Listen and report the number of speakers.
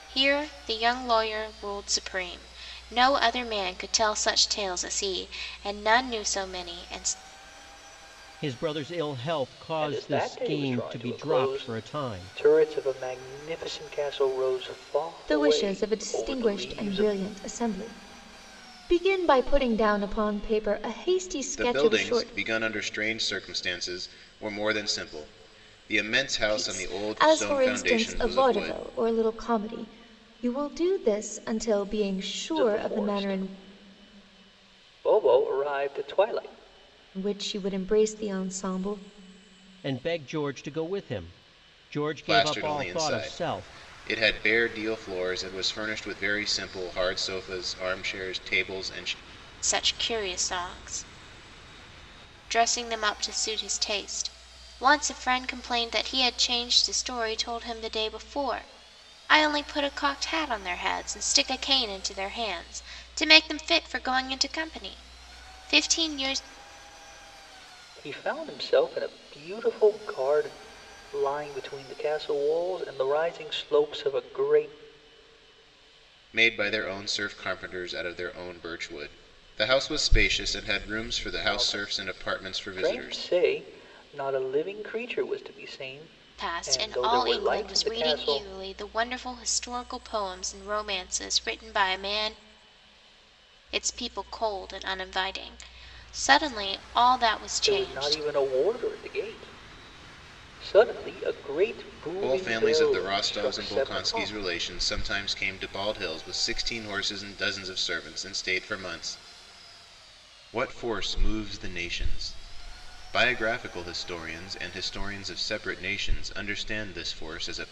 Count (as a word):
five